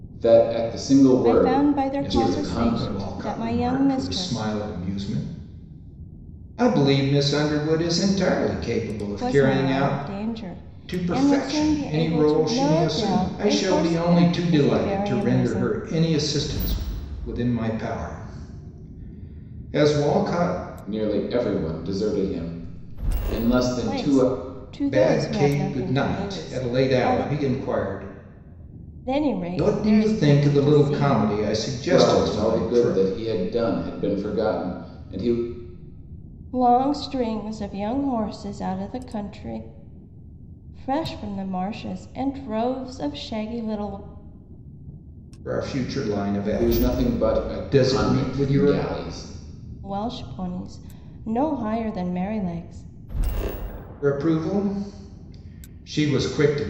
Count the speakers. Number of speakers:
3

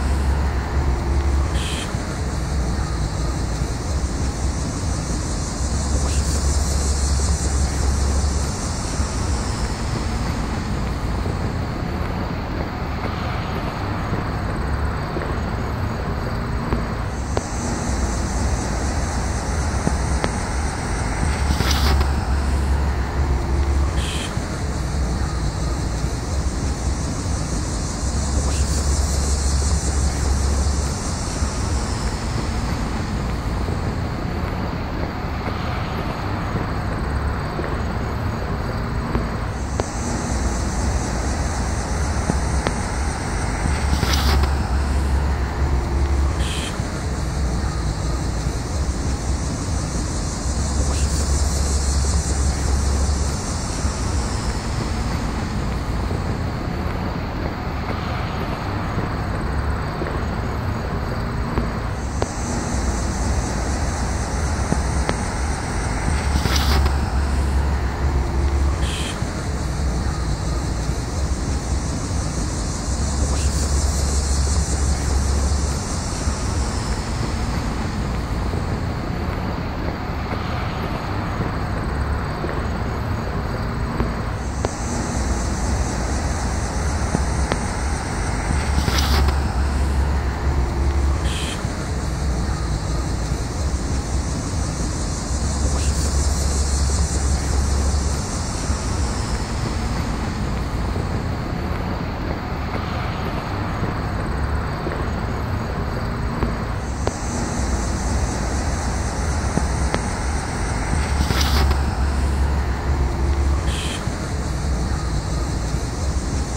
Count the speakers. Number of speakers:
0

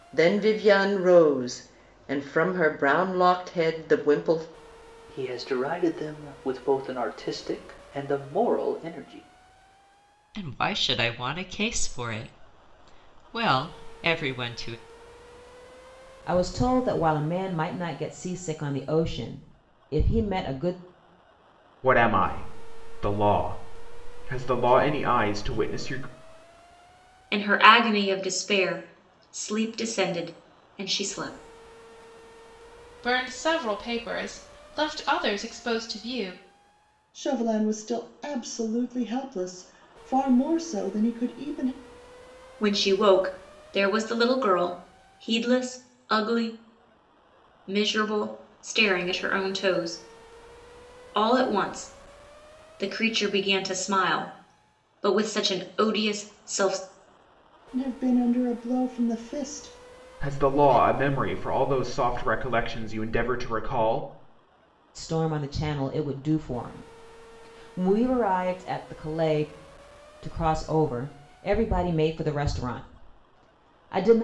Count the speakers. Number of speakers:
8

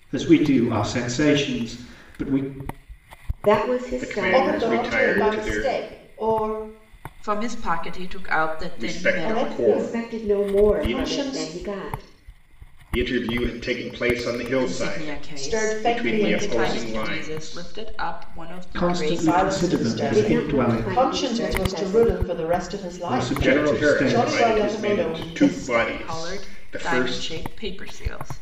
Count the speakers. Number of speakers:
5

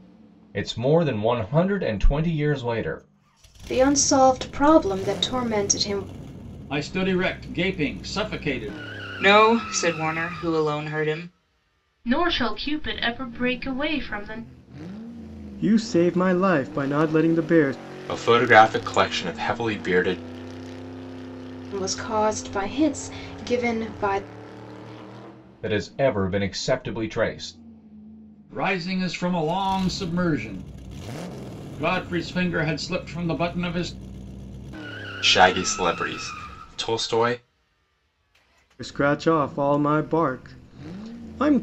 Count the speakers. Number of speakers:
7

